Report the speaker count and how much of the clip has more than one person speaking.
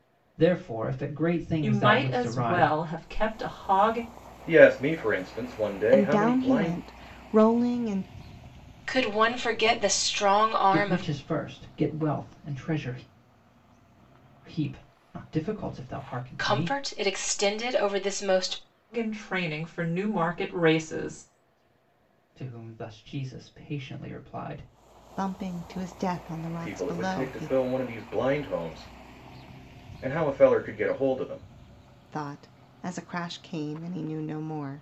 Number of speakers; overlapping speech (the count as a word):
five, about 12%